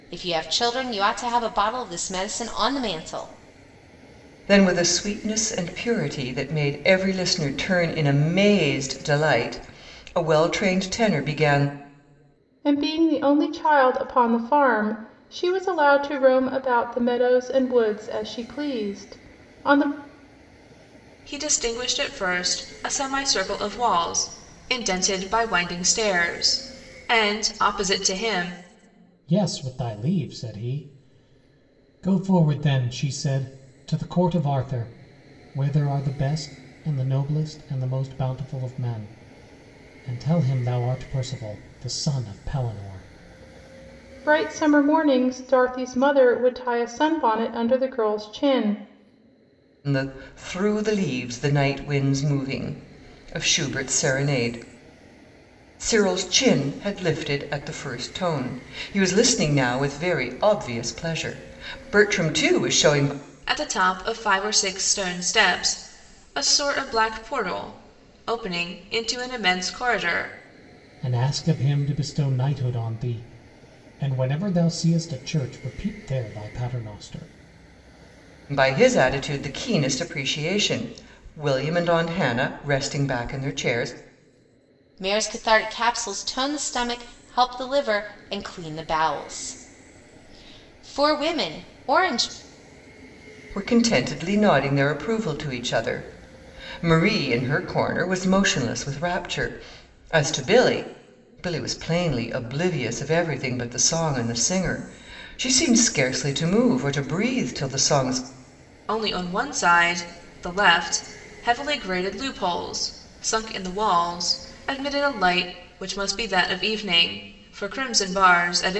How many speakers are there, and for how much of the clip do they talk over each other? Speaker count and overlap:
5, no overlap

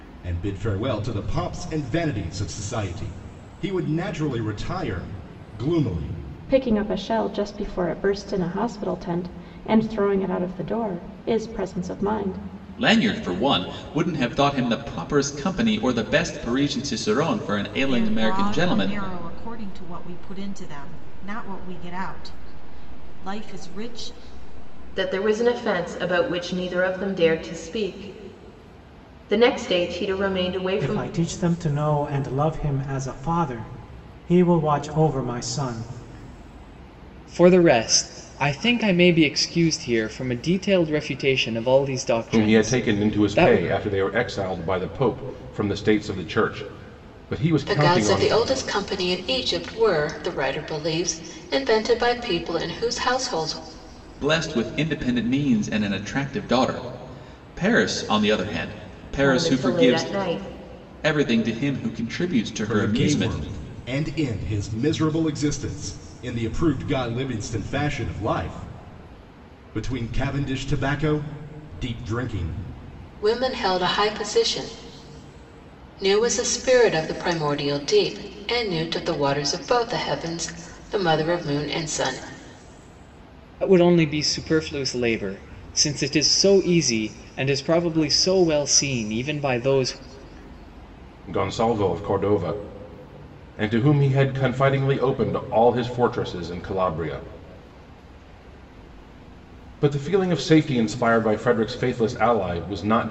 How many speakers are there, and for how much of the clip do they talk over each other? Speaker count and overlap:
9, about 5%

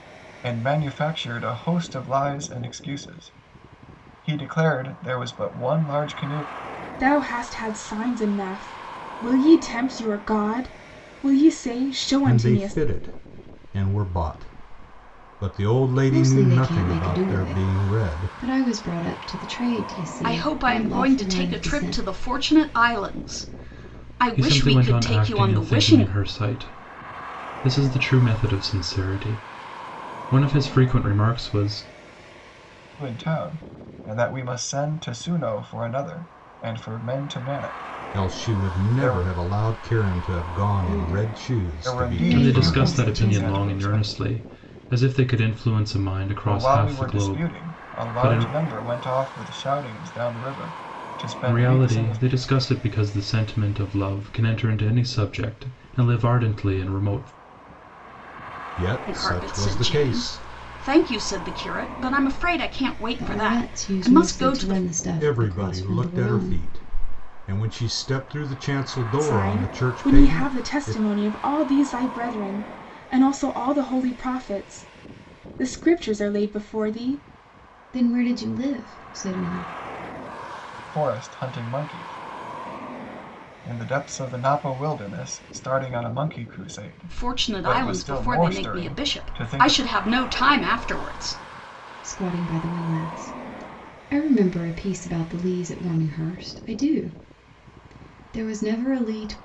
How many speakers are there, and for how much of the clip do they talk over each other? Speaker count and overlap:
6, about 23%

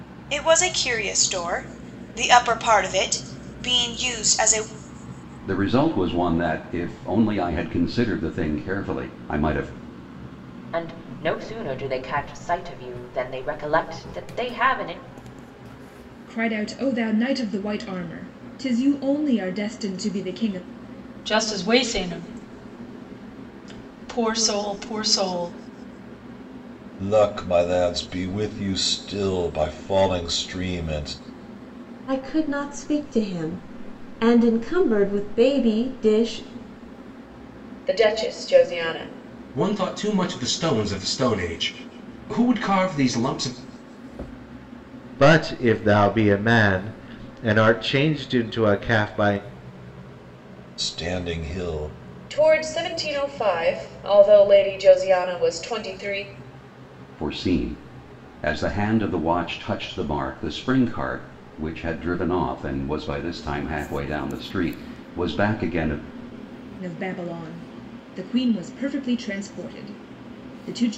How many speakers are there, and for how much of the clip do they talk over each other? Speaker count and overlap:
10, no overlap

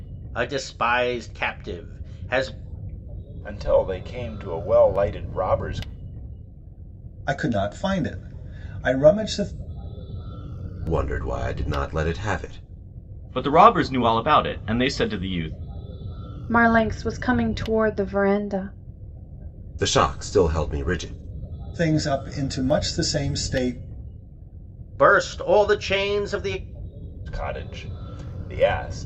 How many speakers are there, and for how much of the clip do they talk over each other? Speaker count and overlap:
6, no overlap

